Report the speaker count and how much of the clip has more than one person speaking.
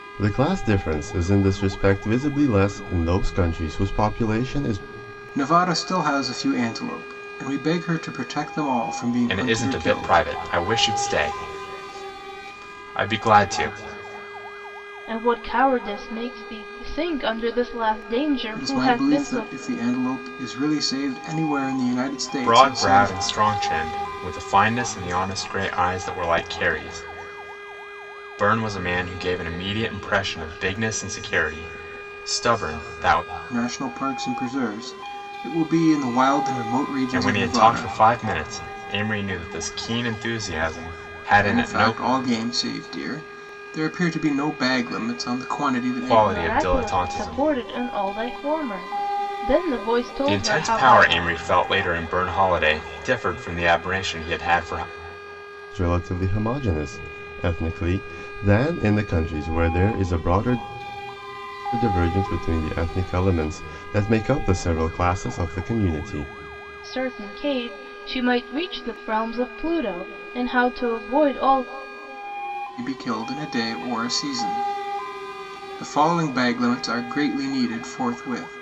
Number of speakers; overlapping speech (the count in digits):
4, about 9%